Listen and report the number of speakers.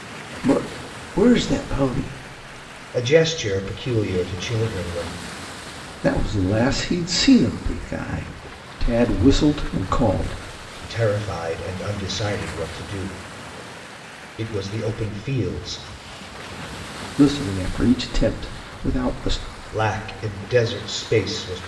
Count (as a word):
two